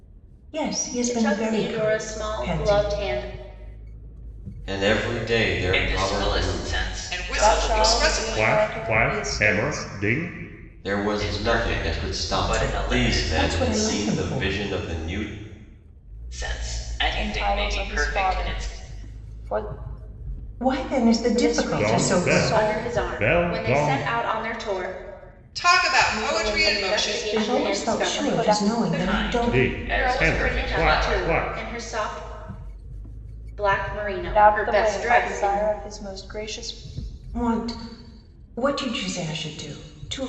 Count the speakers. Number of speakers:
7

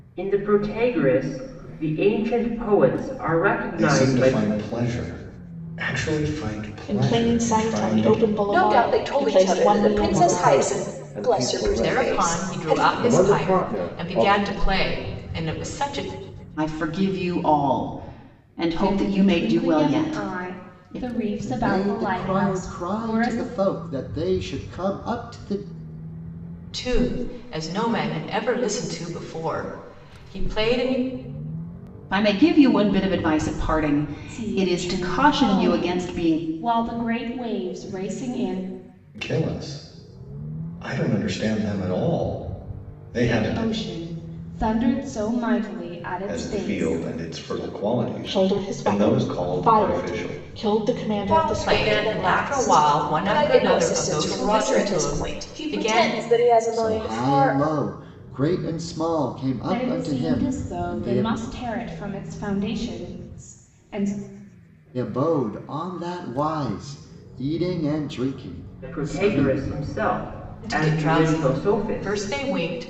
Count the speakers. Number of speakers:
9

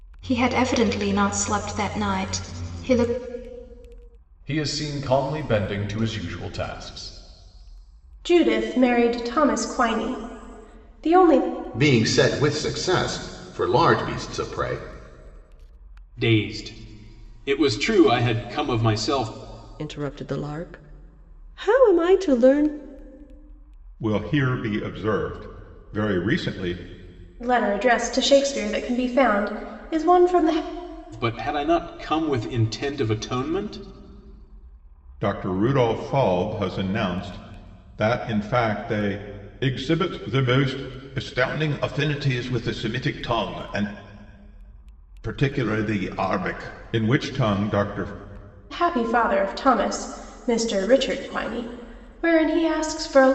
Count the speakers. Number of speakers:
7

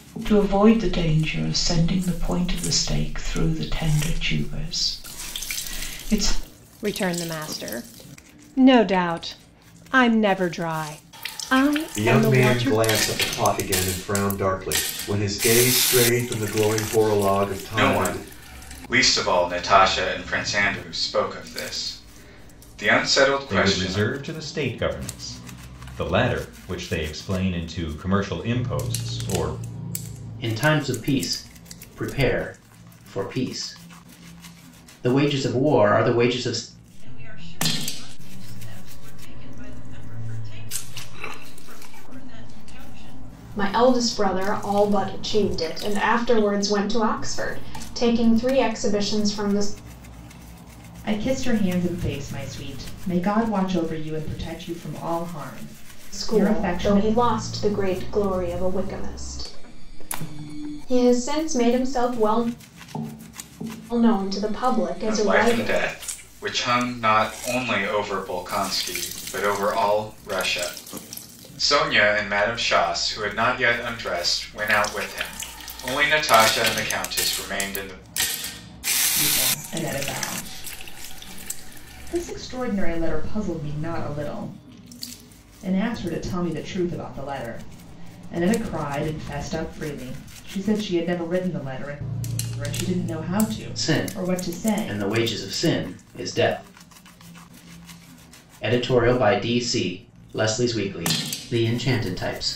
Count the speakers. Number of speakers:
9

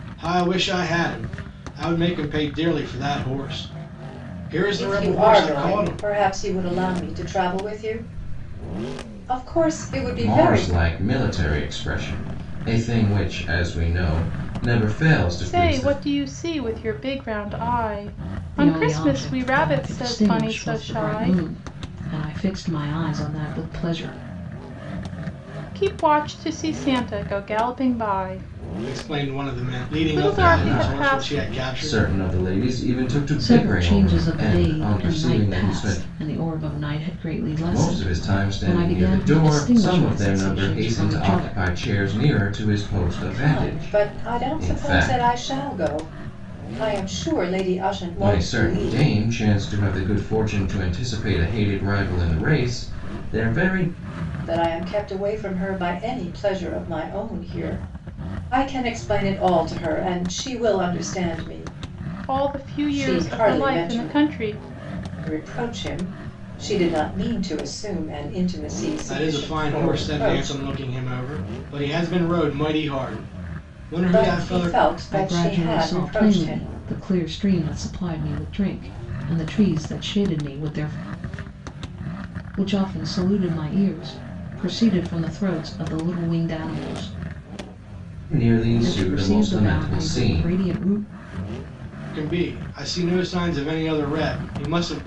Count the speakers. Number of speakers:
5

